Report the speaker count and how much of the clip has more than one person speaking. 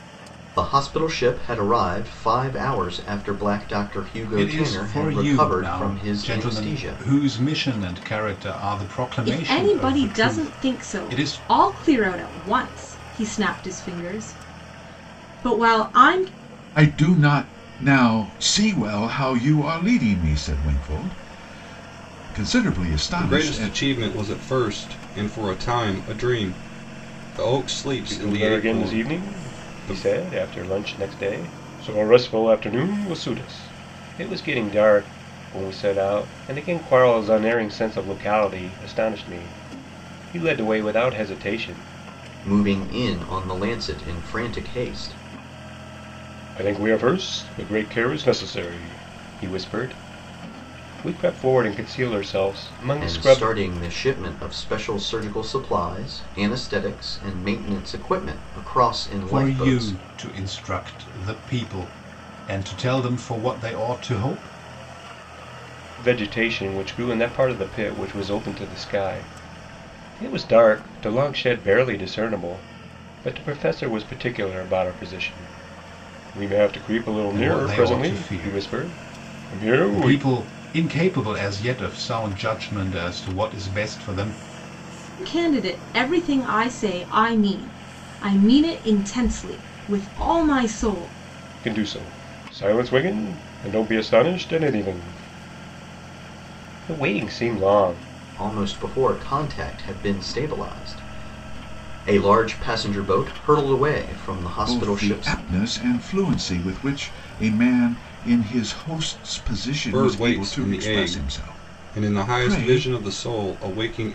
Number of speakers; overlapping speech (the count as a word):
six, about 14%